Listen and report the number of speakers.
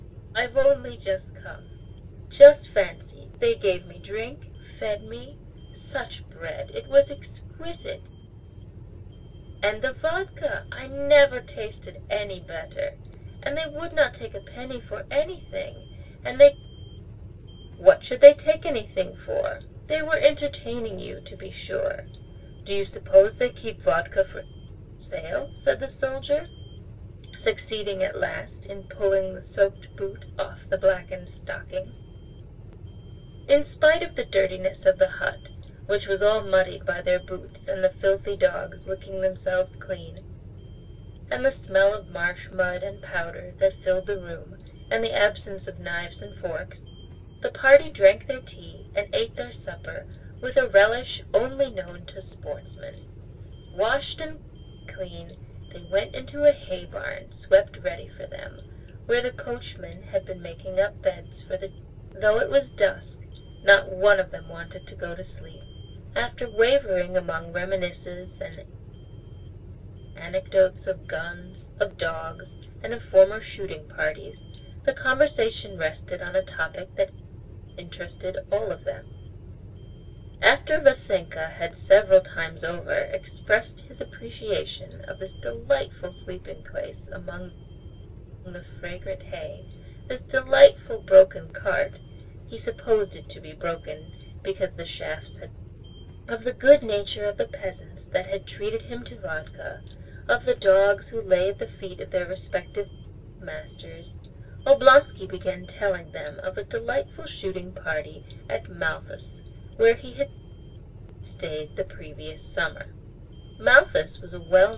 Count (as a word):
one